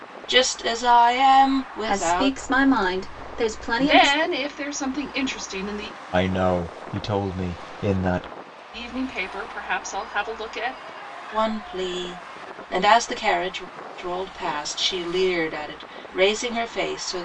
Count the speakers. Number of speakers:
four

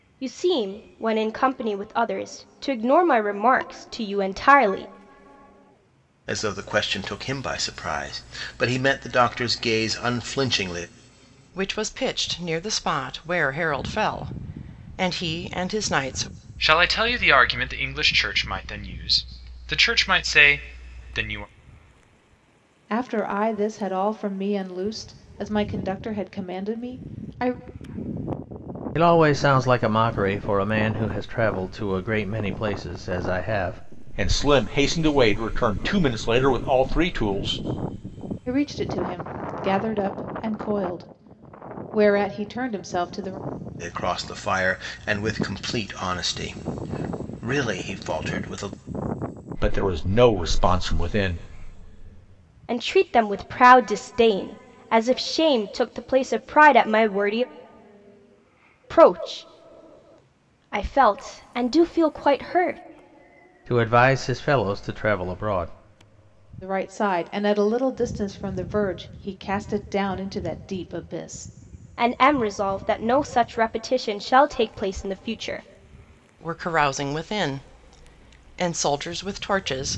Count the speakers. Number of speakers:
seven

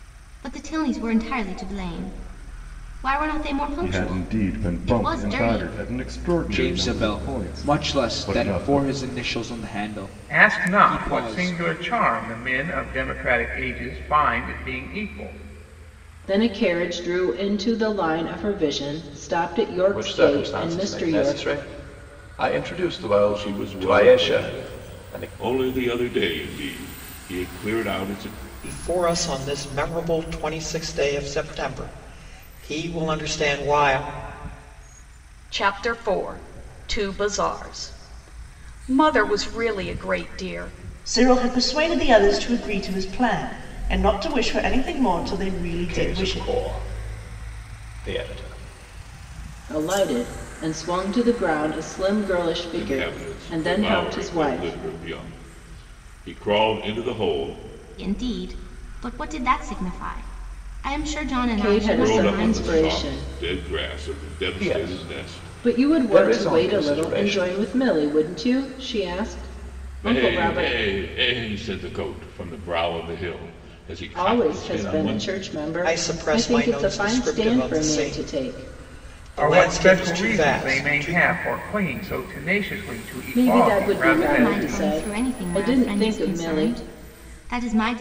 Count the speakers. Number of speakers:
ten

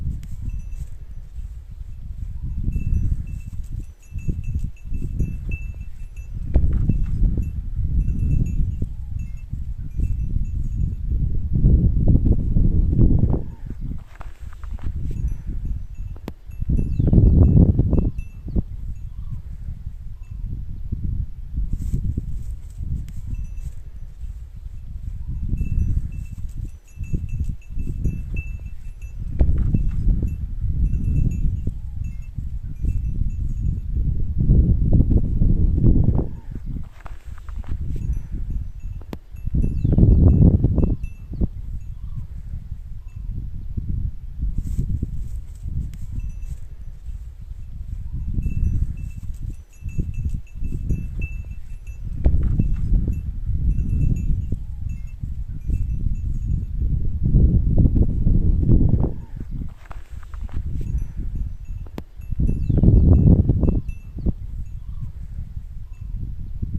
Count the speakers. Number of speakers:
zero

